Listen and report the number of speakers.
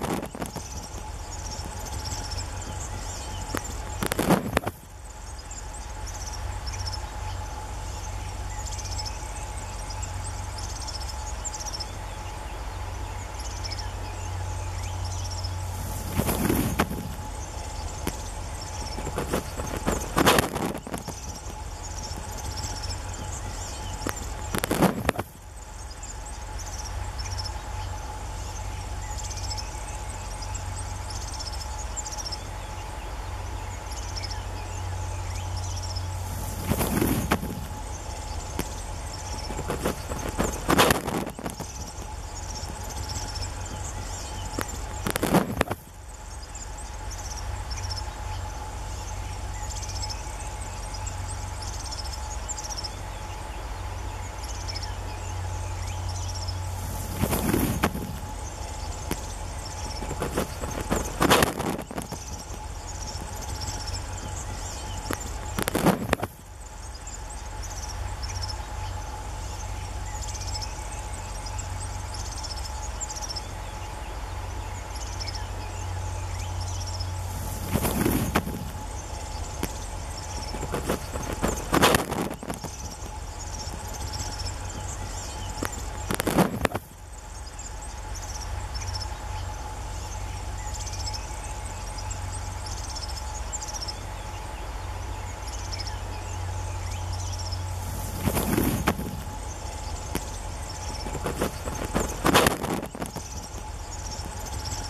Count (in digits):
0